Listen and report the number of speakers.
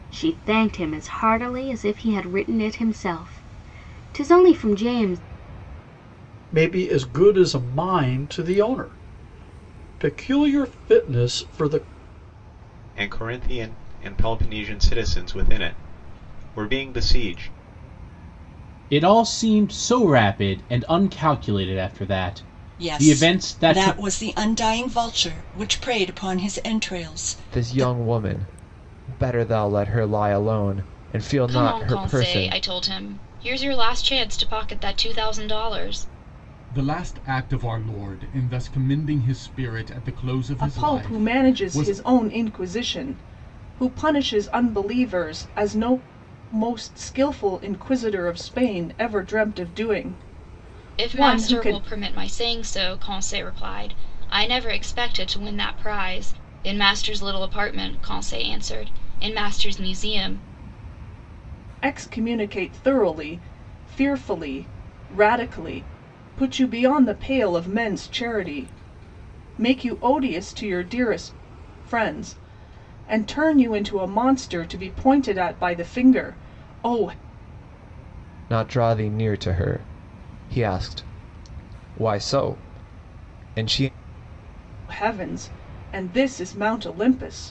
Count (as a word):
nine